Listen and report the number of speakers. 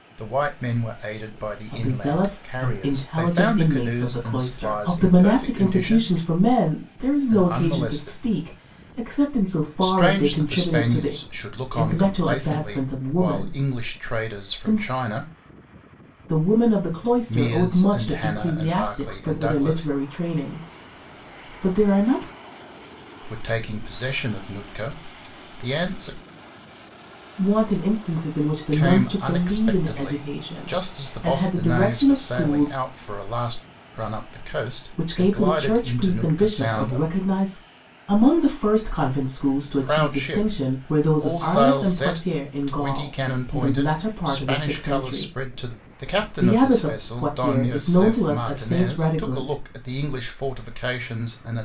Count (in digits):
2